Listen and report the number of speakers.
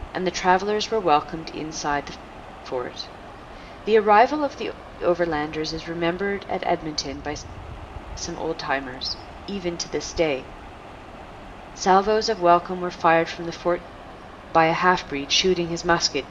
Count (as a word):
one